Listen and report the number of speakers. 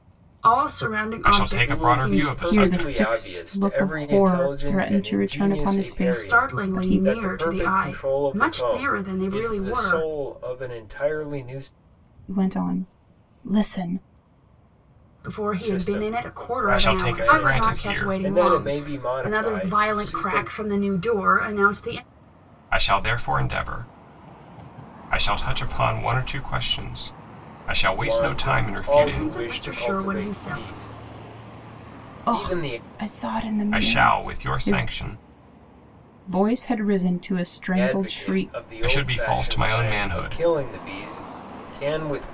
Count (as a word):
four